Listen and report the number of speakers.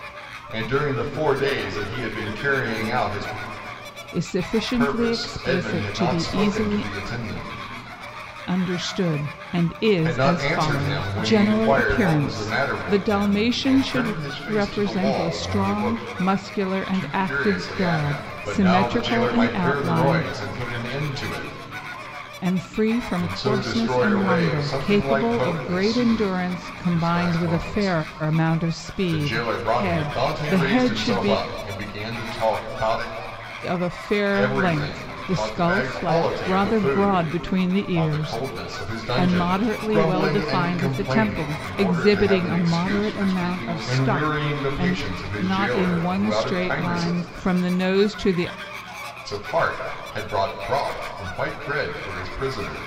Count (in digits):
2